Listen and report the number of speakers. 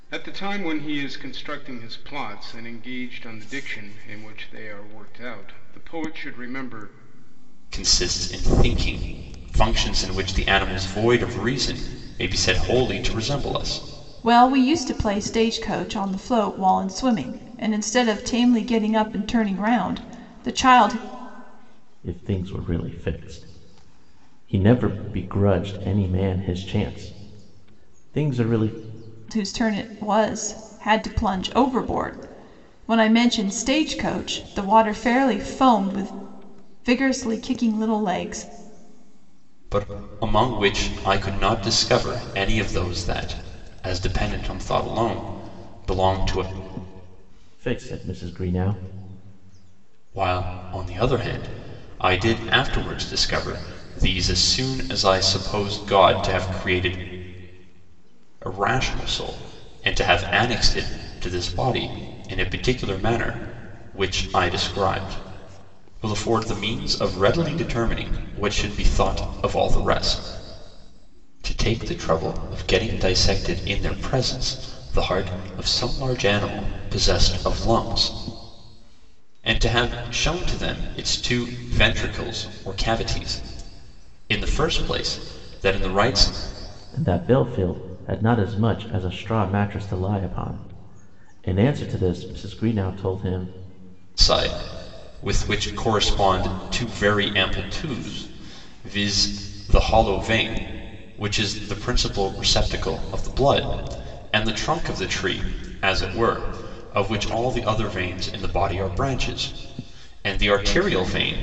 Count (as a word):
four